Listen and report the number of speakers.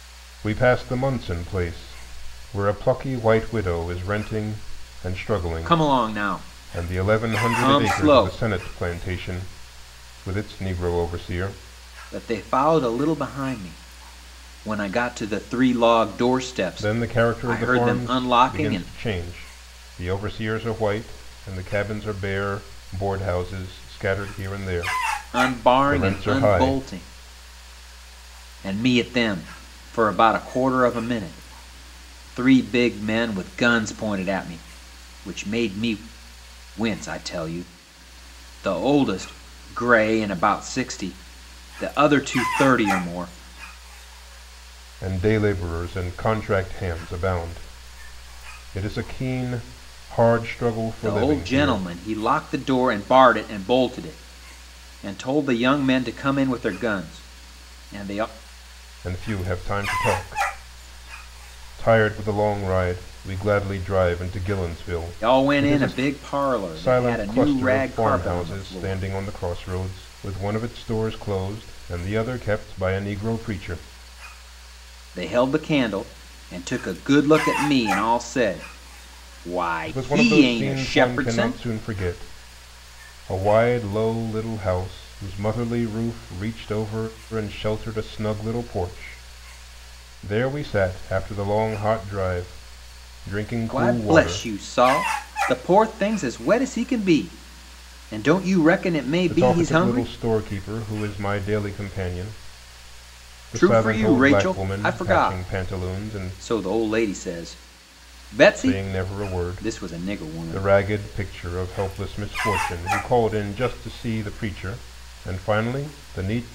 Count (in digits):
2